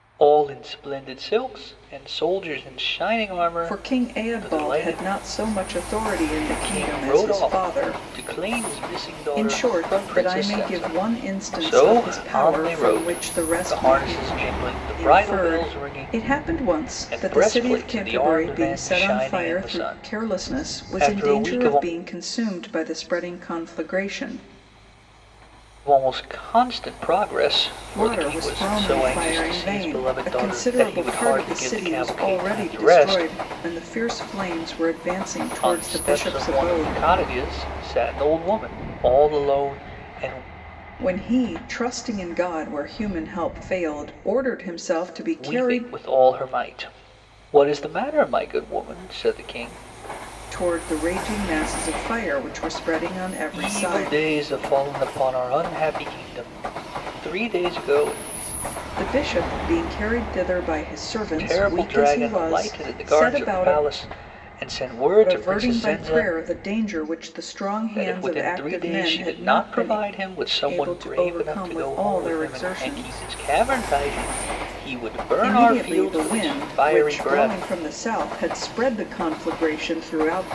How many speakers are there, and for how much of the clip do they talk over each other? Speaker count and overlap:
2, about 39%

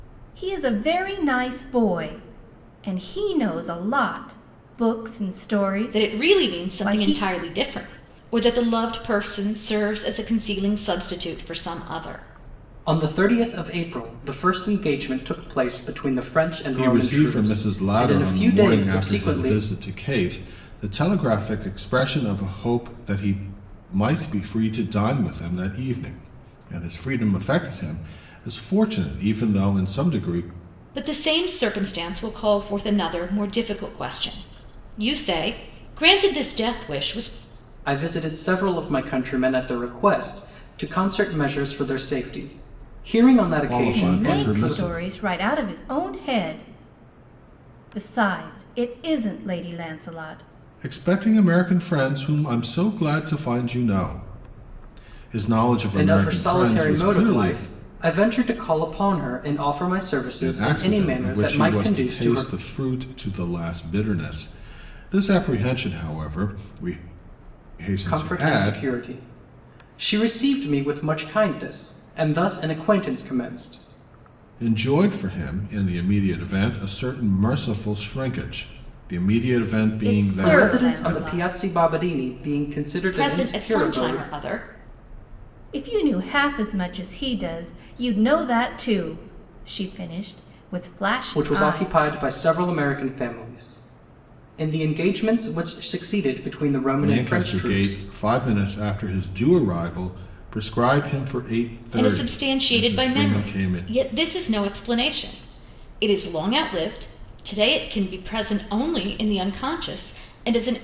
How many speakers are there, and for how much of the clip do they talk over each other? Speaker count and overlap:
4, about 15%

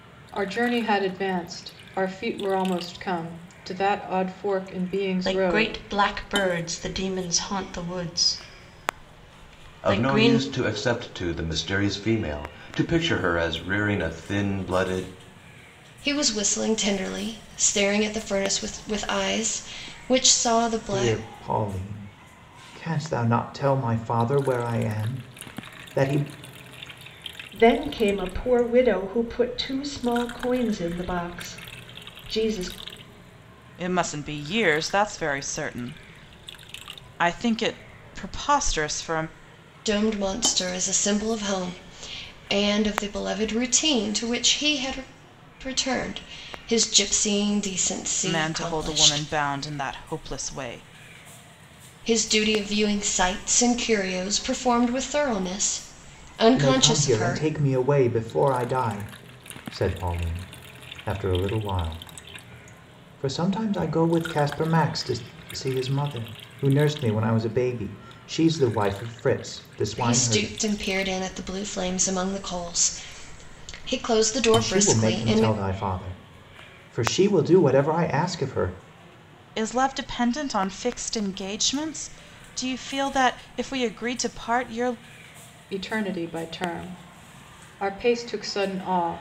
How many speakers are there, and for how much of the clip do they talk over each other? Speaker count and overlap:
7, about 6%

